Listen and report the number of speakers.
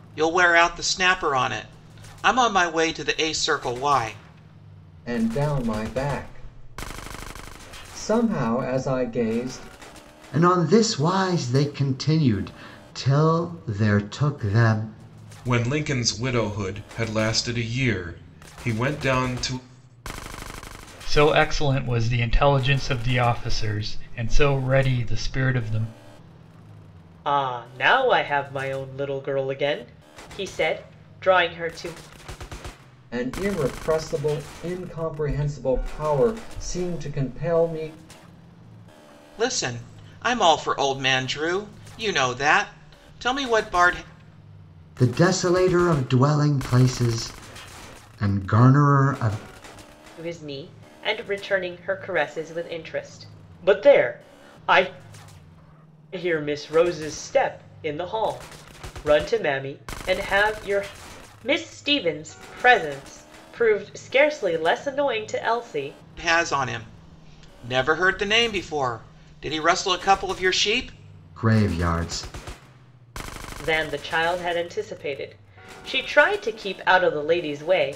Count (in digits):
6